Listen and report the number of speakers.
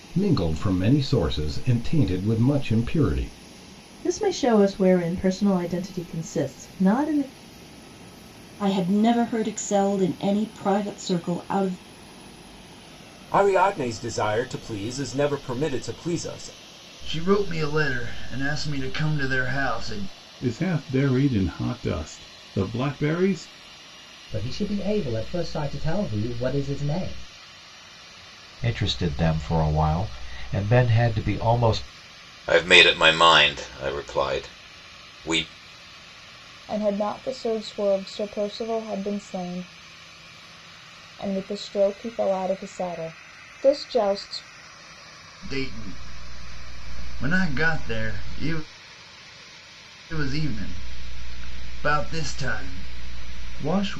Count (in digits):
10